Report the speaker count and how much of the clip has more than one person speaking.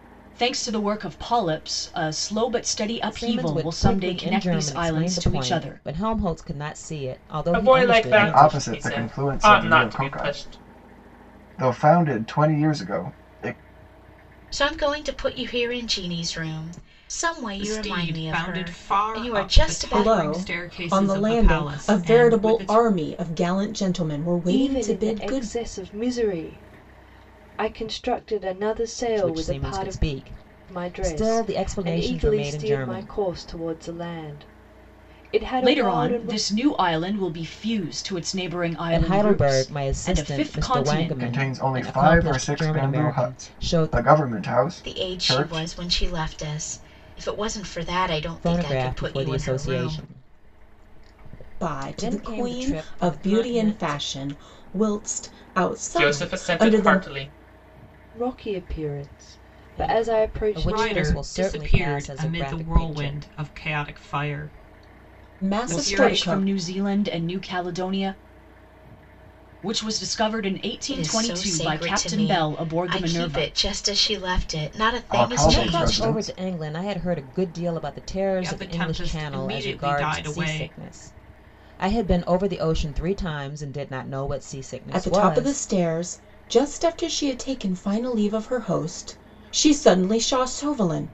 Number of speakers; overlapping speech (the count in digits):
8, about 43%